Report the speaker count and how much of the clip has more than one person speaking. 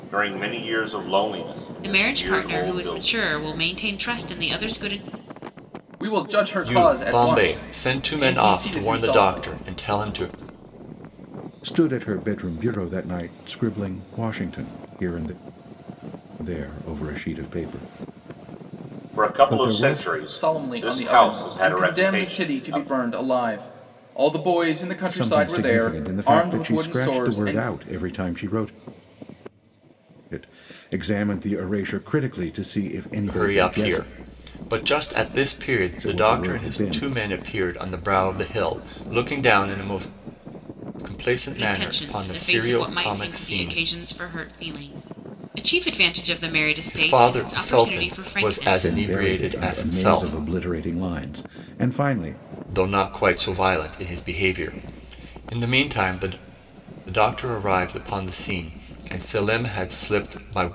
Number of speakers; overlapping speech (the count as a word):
five, about 30%